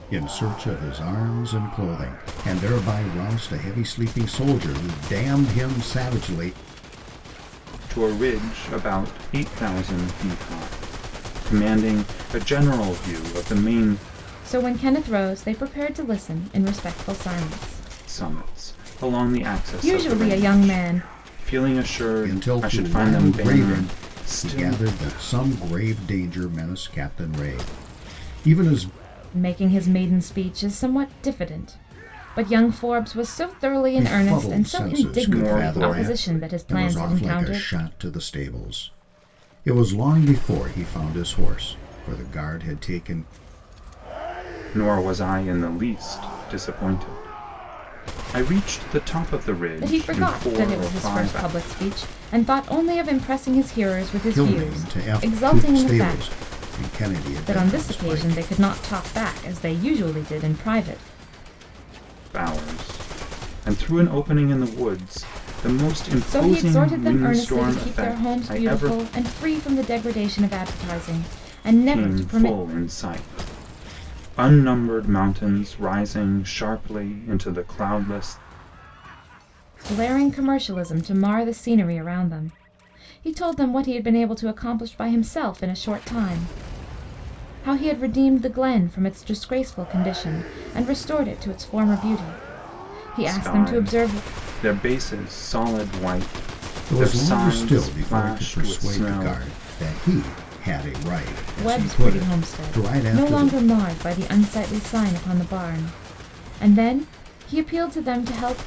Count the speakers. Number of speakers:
3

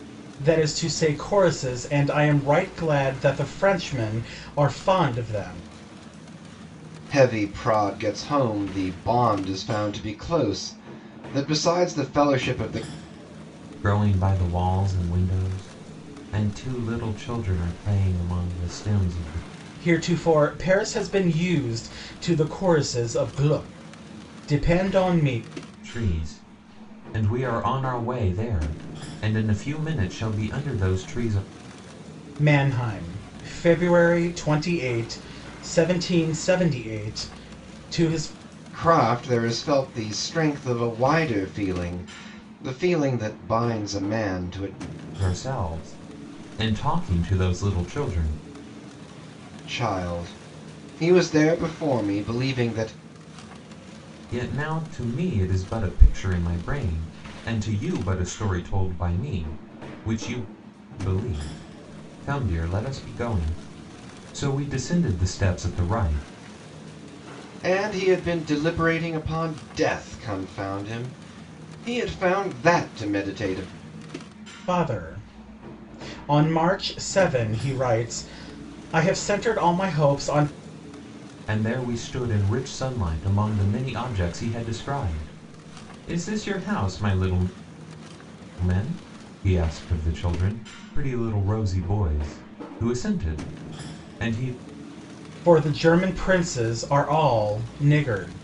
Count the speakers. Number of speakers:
3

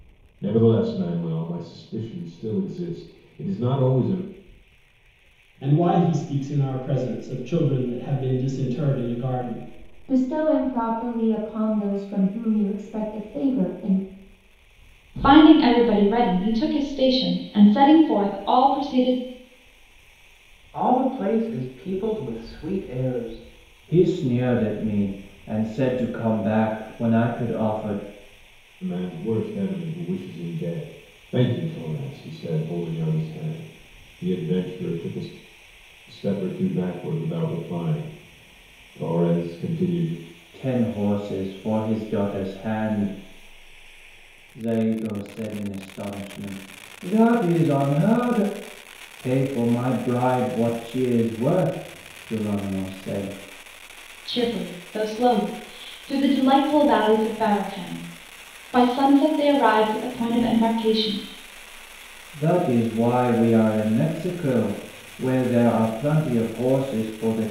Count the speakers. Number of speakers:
6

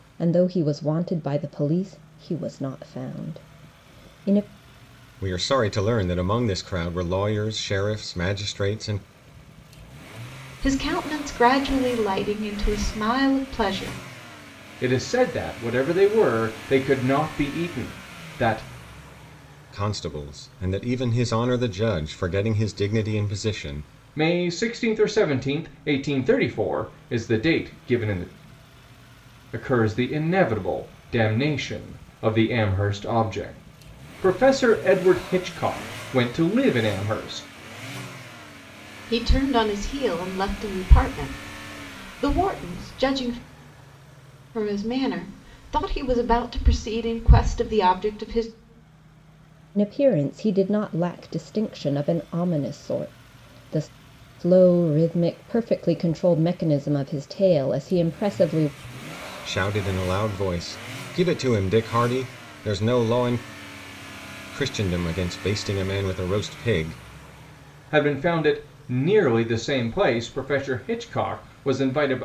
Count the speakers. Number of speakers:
4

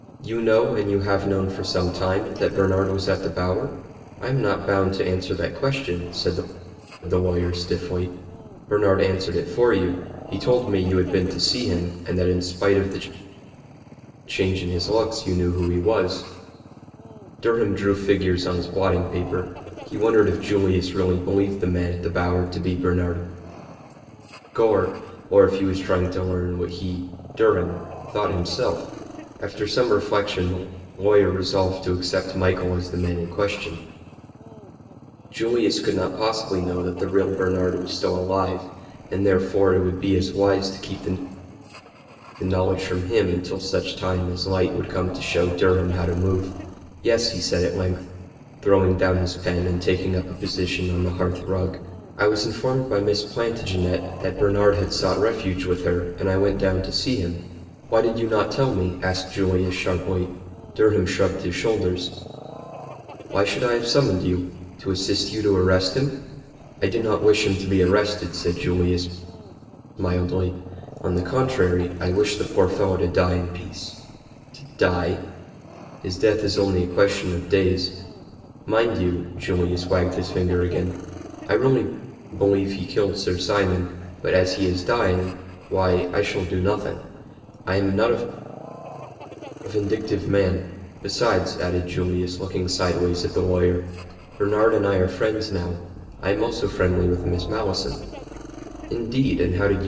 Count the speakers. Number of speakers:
1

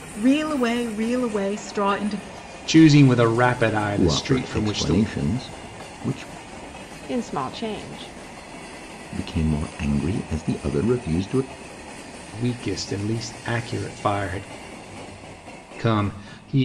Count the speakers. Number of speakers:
4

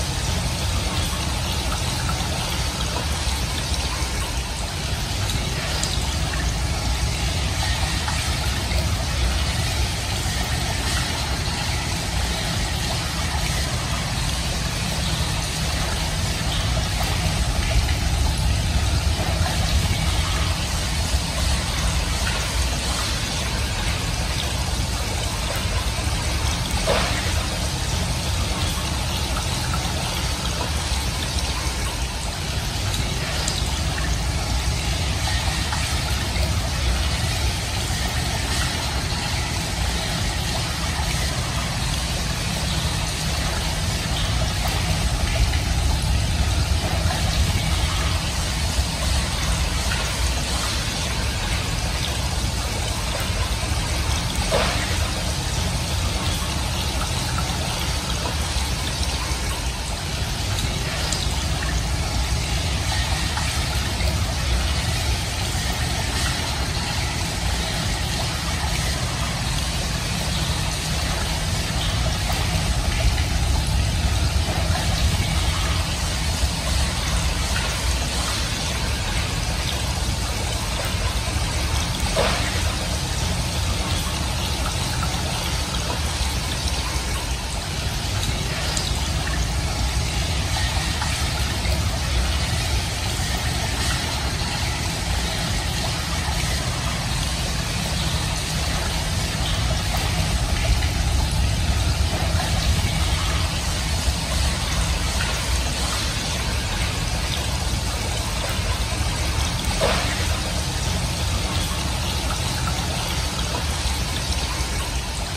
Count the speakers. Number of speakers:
0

